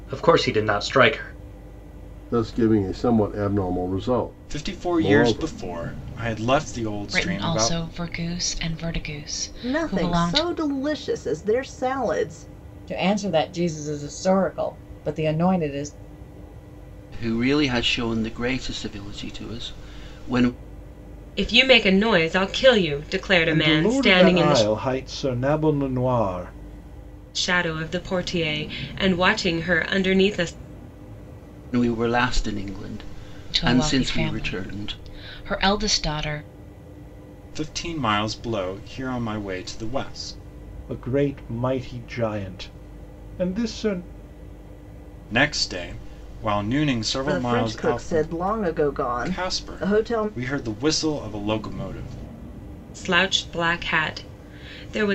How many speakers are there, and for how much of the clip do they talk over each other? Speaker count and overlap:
9, about 14%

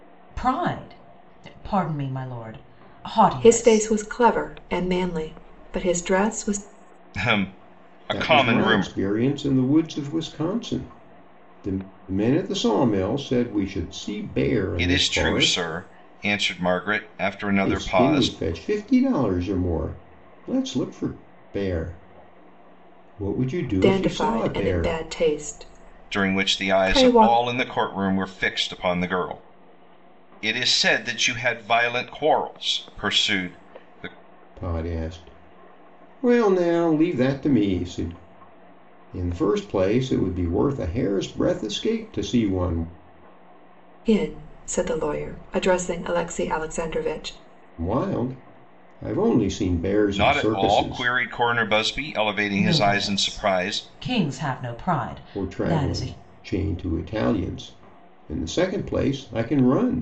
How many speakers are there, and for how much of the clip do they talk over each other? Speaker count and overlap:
4, about 15%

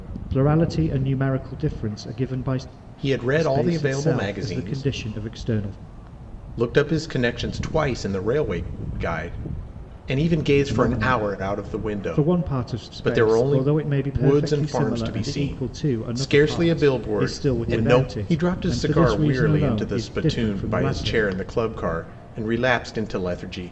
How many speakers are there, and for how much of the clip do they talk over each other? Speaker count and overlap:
2, about 47%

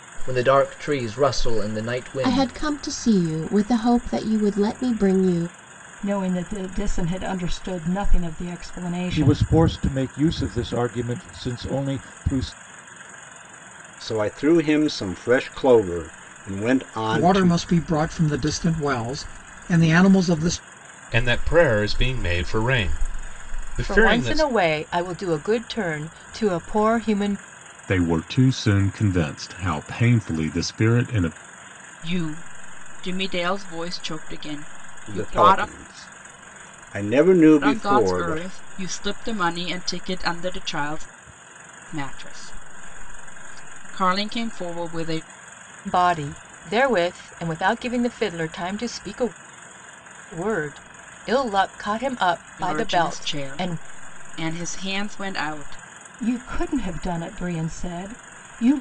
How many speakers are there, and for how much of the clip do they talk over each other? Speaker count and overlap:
10, about 8%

